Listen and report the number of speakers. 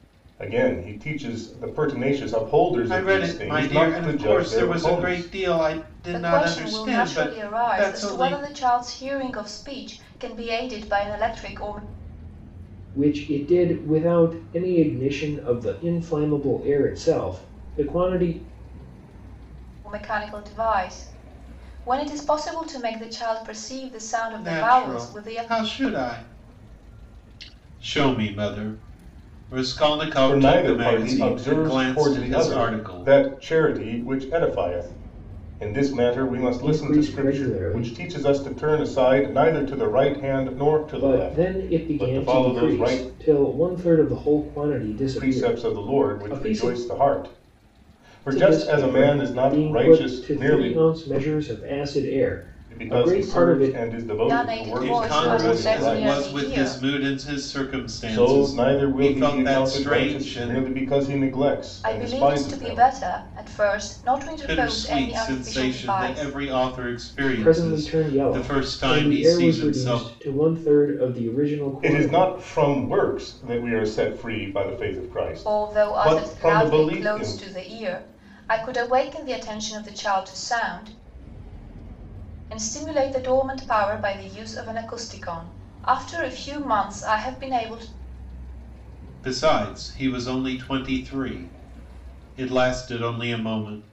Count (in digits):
4